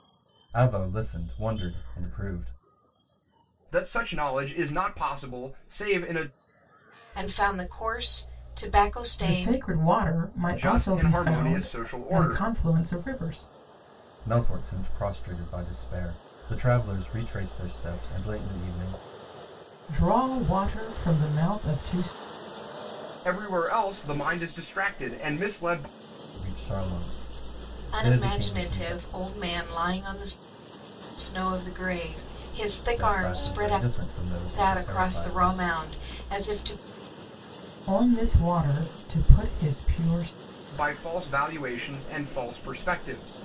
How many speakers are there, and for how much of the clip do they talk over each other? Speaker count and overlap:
4, about 12%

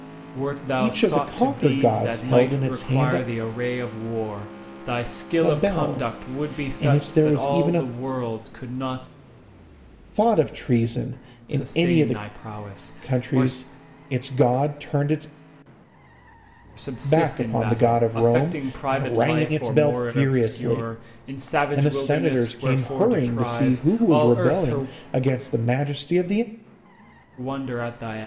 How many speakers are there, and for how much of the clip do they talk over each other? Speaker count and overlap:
2, about 47%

